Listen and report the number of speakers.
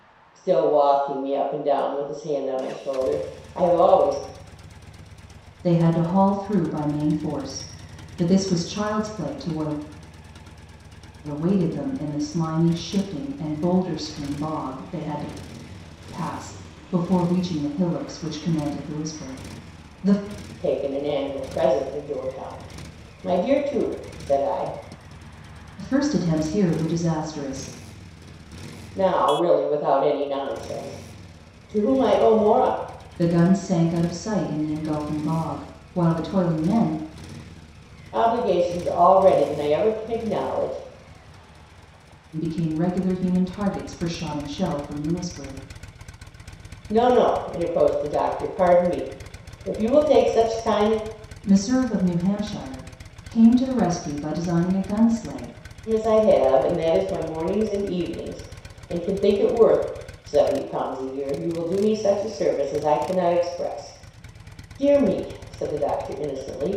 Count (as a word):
two